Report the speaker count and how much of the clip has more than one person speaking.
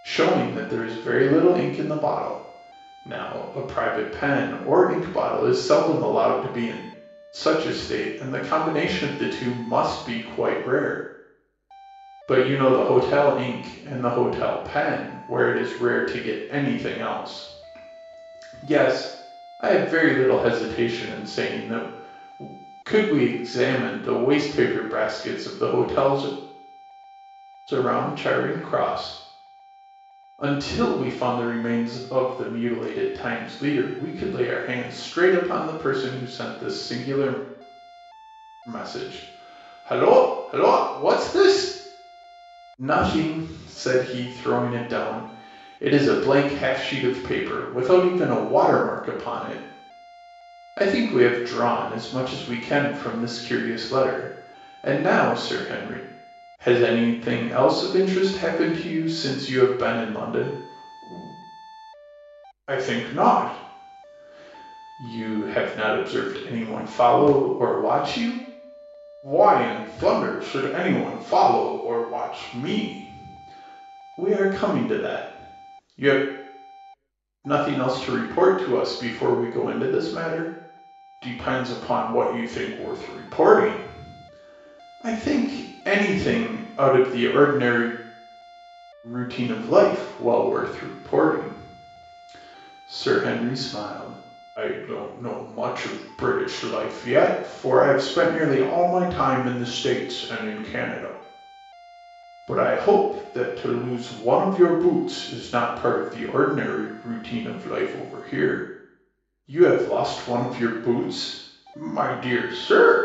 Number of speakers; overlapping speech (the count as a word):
one, no overlap